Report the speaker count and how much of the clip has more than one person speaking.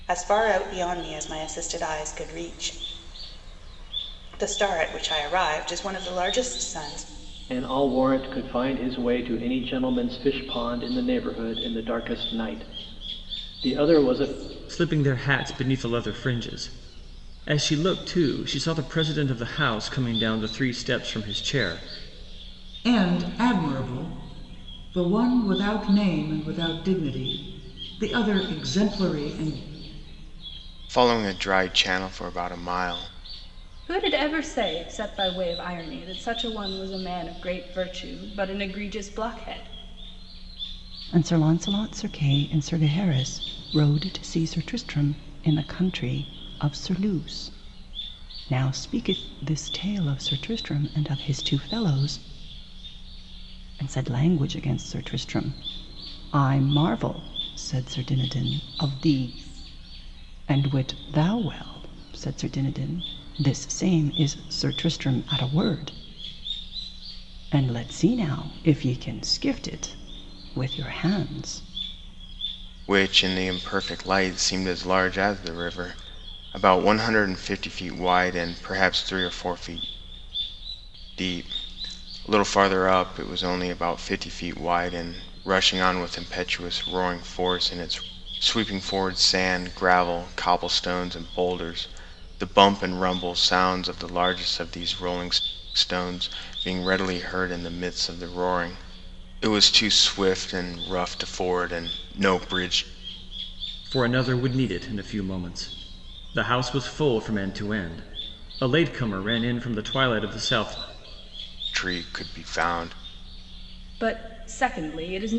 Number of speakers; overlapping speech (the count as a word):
seven, no overlap